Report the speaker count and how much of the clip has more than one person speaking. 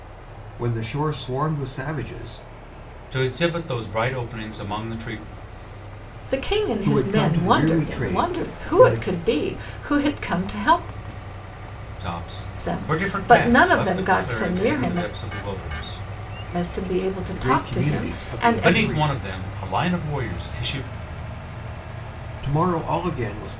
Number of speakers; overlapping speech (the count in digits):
3, about 28%